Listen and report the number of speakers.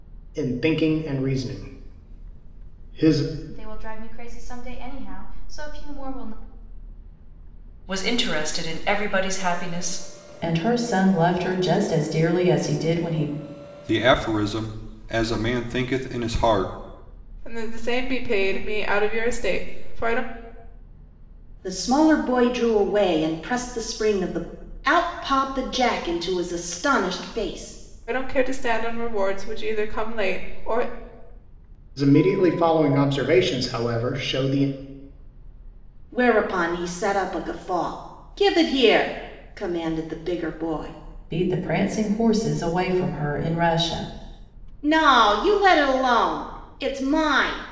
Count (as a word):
seven